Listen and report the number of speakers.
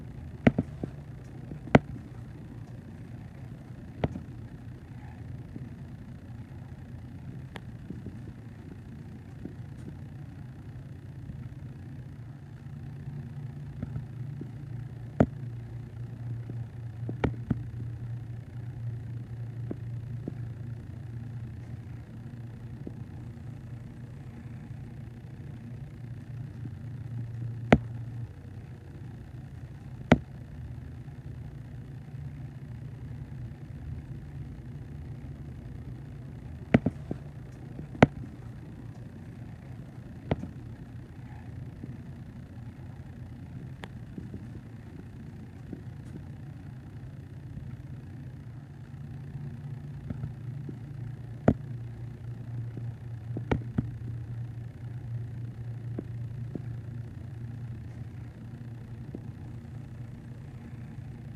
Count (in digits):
0